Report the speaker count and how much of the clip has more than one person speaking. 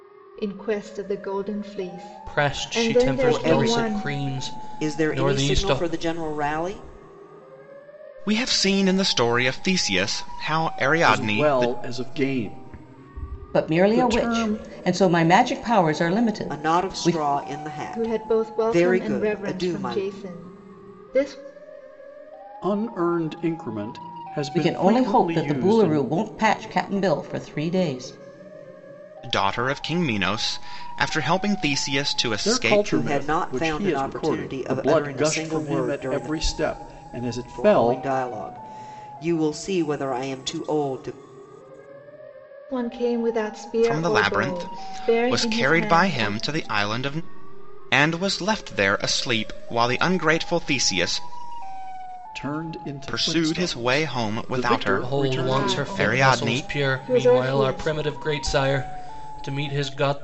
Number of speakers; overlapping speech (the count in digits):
6, about 37%